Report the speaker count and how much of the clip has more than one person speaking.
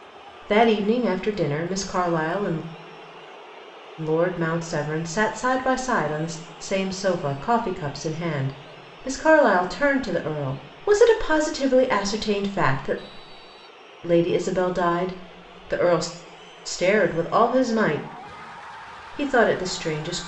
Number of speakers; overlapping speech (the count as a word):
one, no overlap